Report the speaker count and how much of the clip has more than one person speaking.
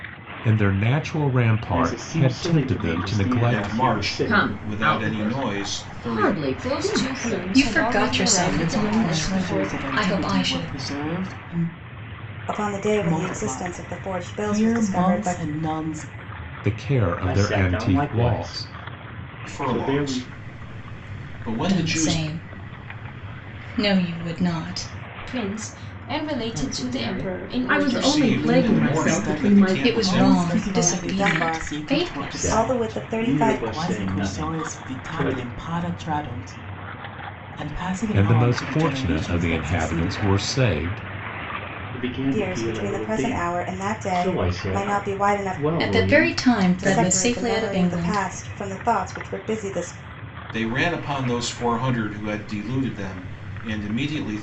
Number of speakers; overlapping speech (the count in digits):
8, about 57%